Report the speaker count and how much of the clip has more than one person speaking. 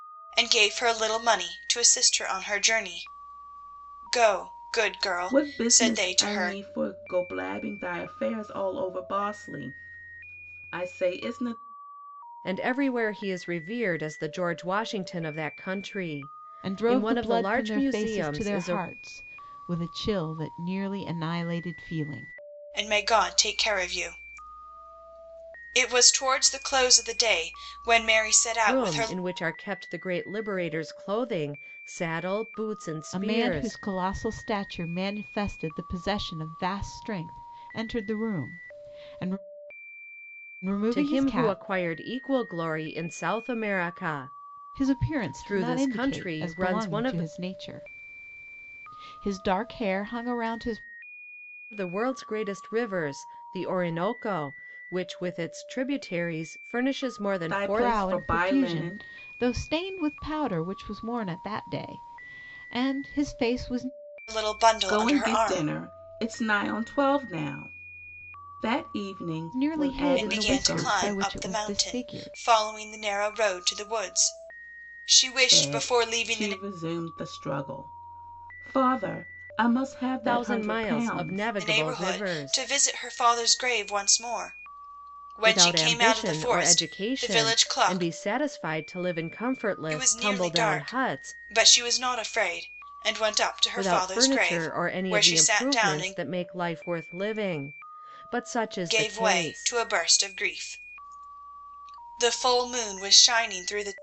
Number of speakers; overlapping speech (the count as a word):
four, about 24%